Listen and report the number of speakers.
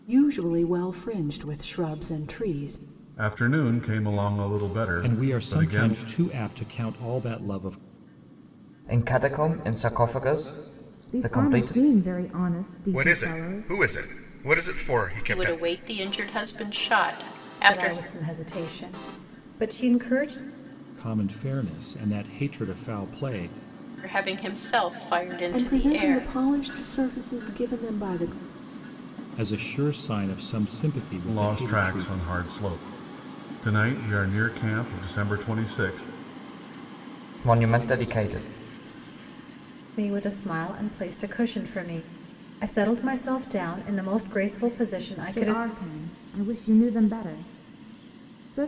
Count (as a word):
eight